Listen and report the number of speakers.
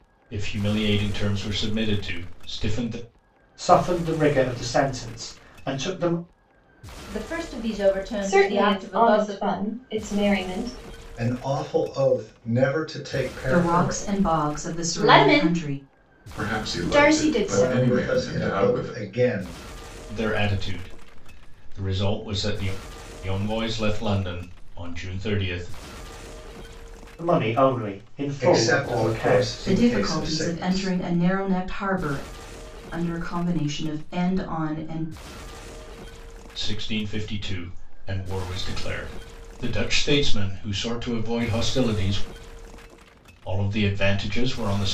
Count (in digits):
8